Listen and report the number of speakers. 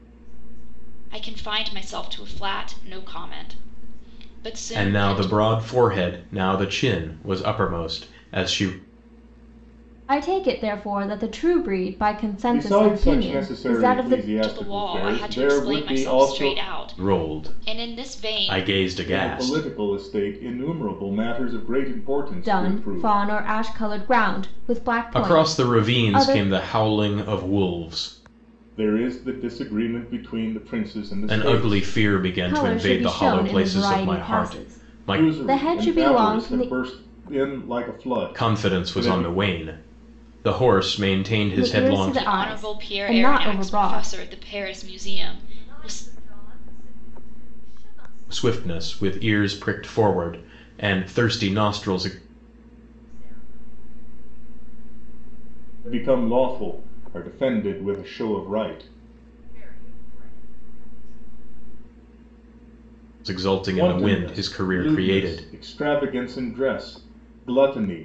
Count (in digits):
5